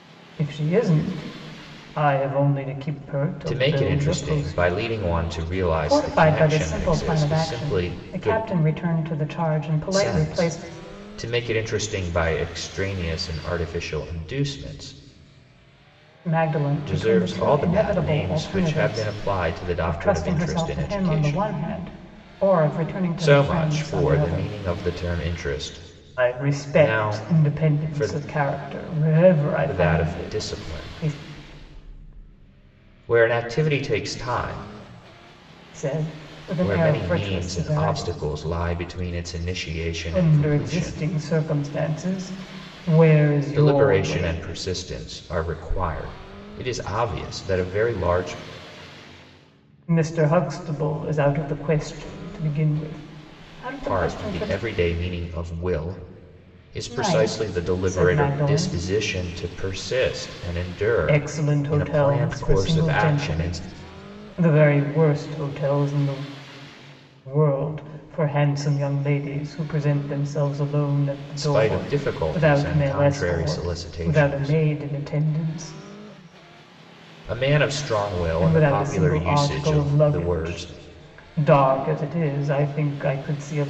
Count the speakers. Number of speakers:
2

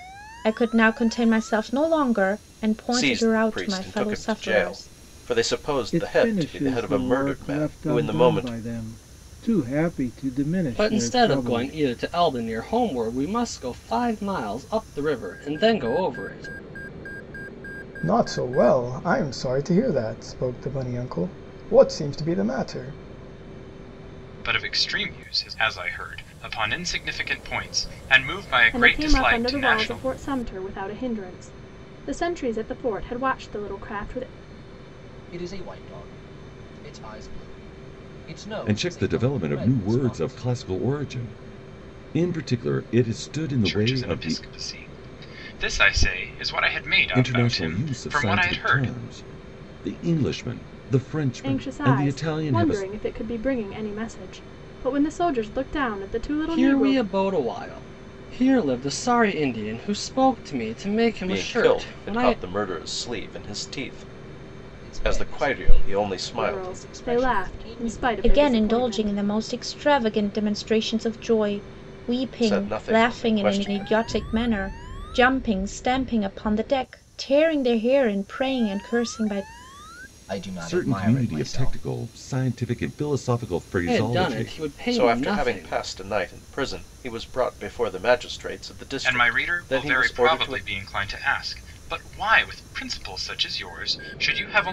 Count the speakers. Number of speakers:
9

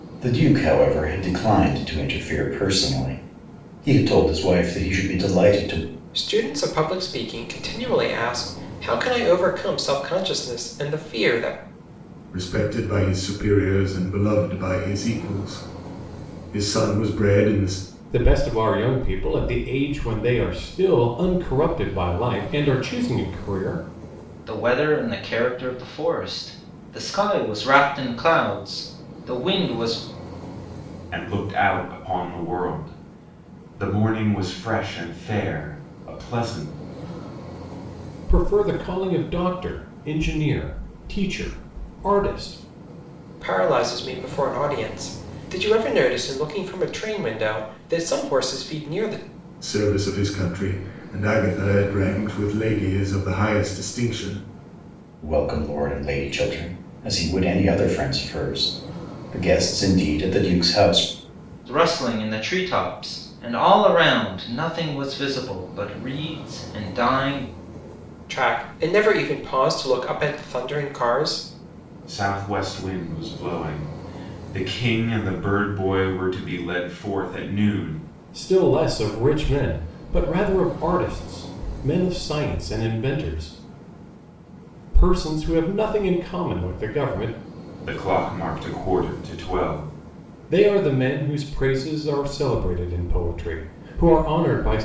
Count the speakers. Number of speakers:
6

